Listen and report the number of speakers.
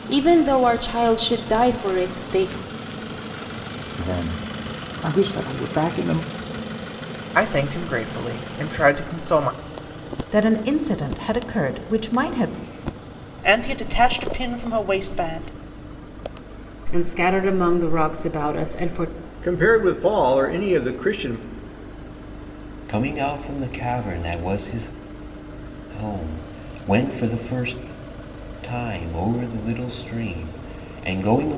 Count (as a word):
eight